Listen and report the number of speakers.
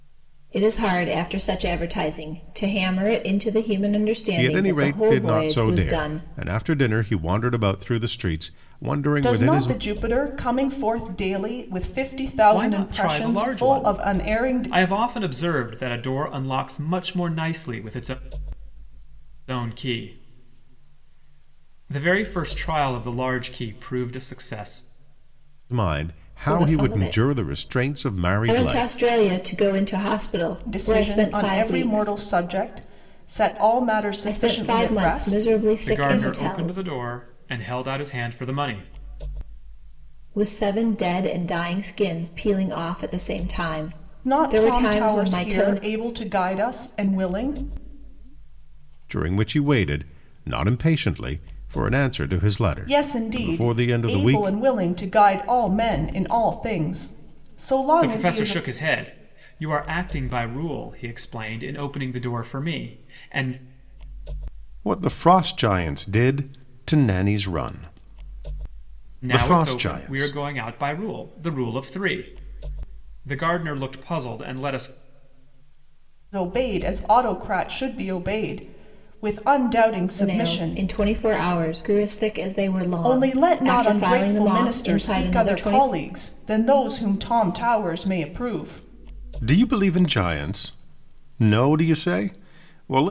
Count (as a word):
four